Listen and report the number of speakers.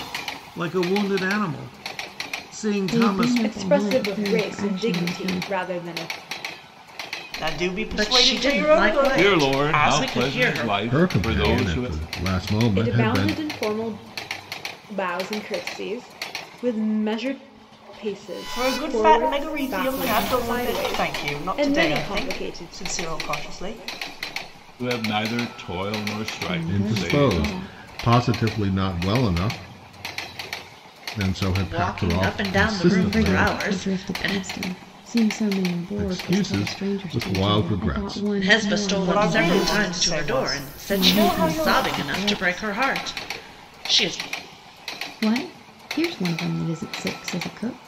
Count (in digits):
7